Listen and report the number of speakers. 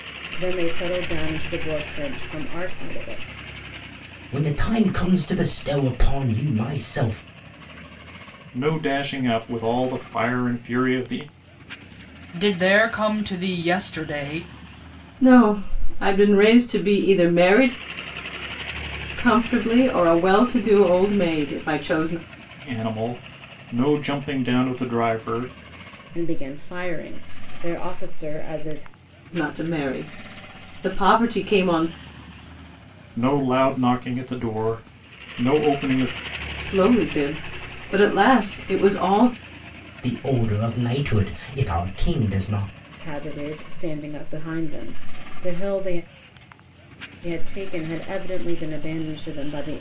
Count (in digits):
5